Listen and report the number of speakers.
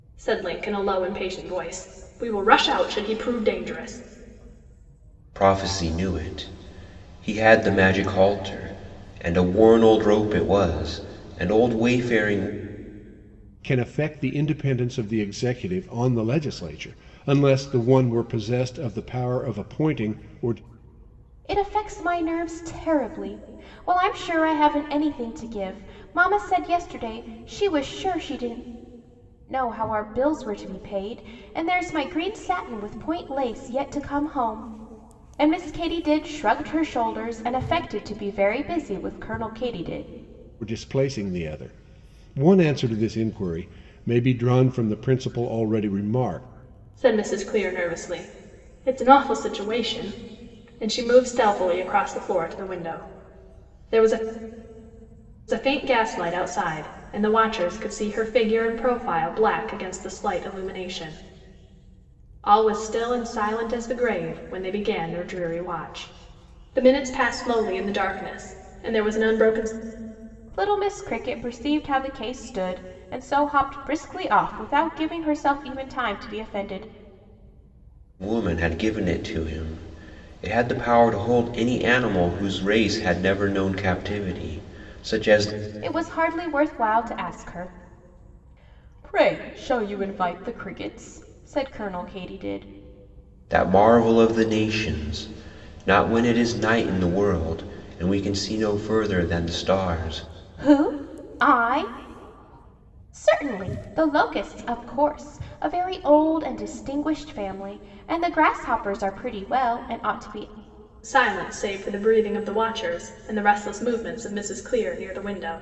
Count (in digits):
4